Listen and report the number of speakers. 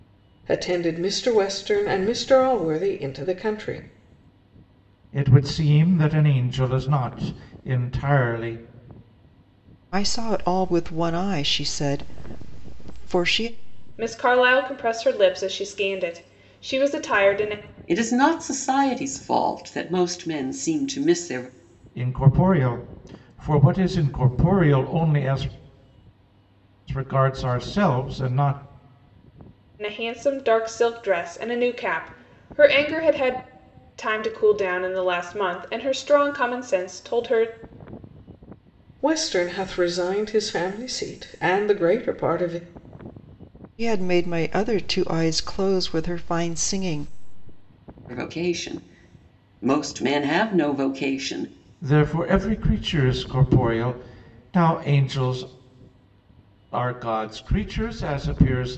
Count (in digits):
5